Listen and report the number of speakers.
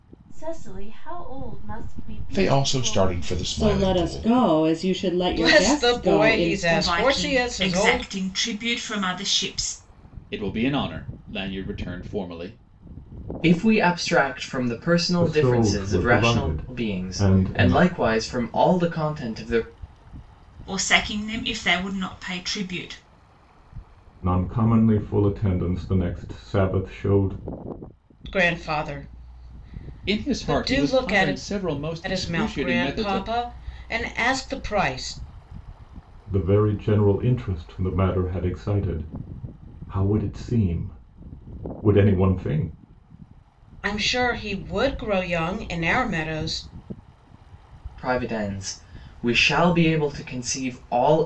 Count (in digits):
8